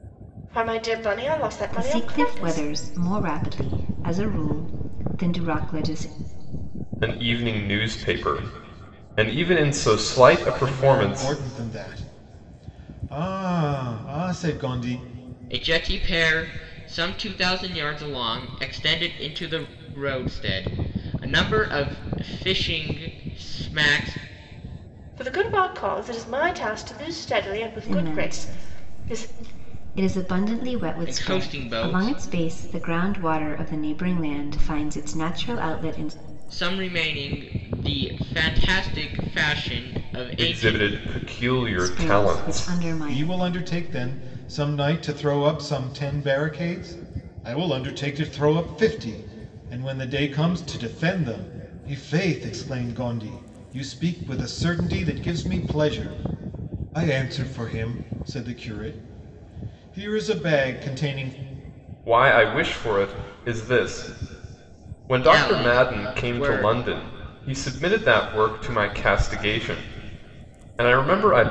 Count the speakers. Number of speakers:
five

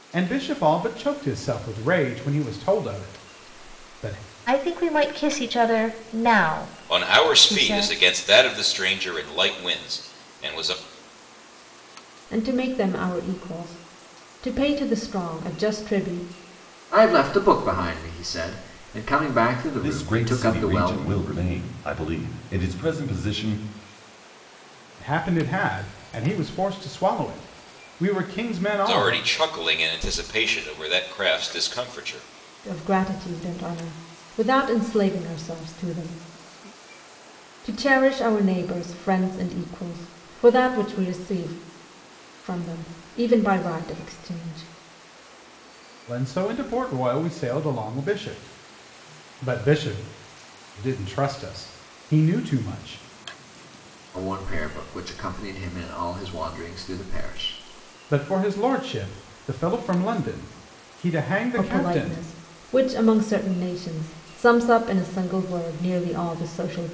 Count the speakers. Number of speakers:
six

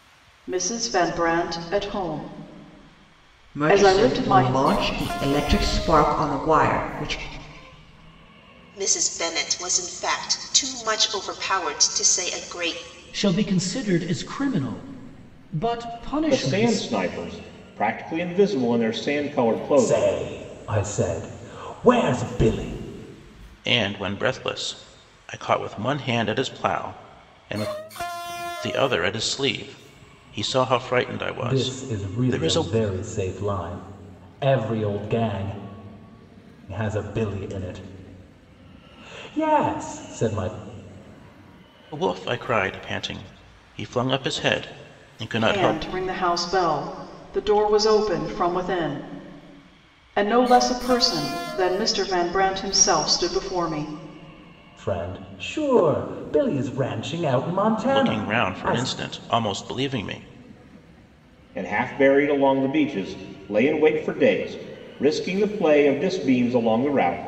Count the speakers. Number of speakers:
seven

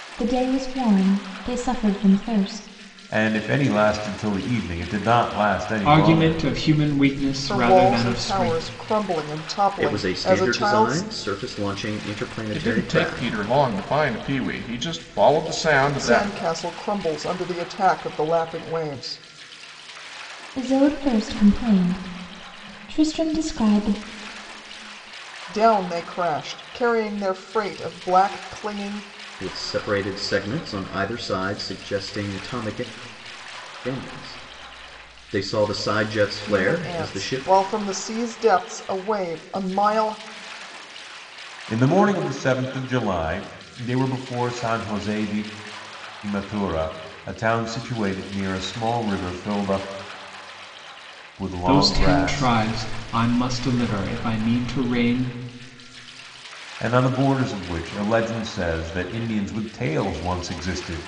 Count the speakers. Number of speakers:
six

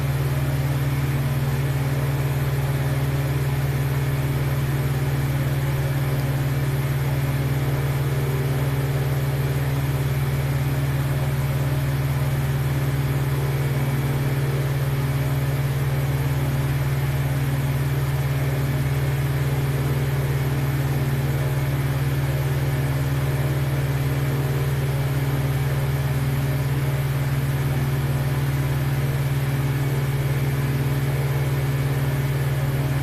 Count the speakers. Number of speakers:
zero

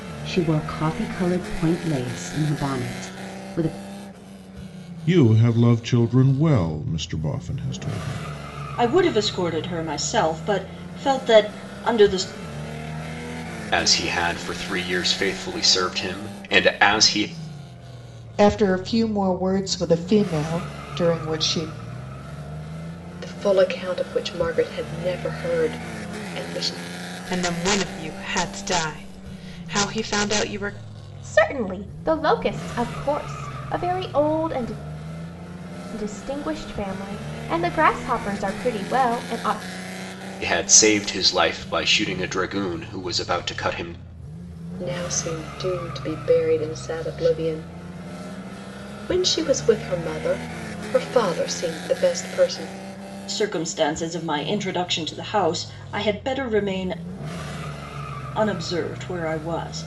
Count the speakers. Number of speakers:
eight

